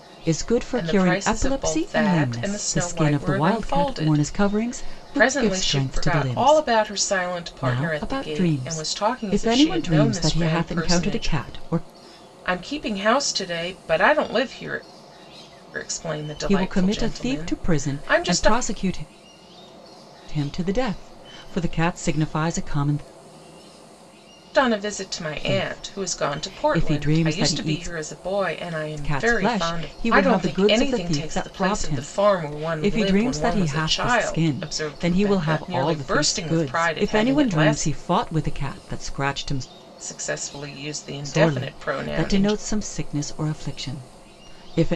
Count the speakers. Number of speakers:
2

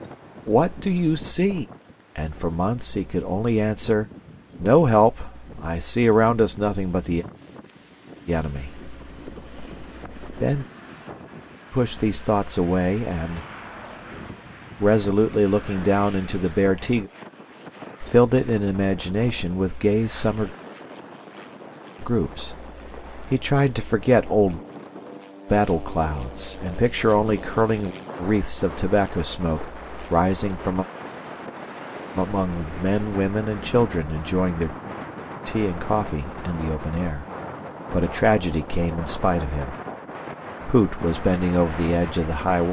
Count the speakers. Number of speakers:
1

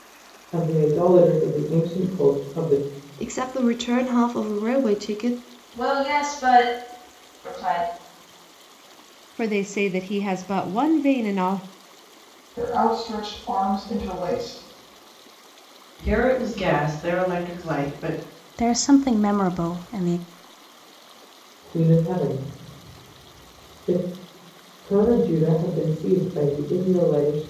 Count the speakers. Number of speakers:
7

